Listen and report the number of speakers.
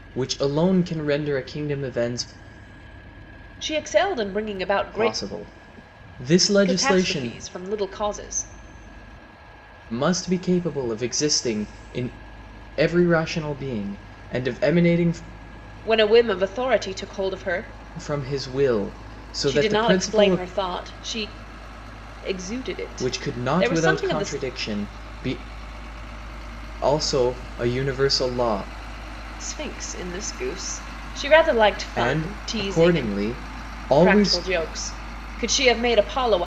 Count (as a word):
two